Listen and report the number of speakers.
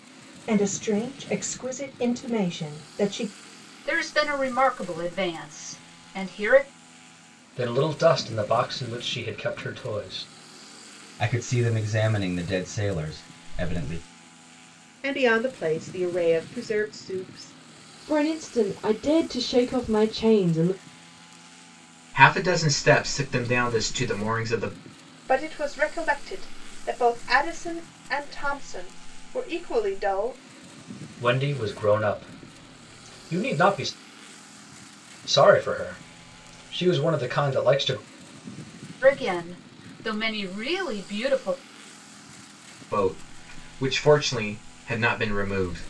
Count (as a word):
eight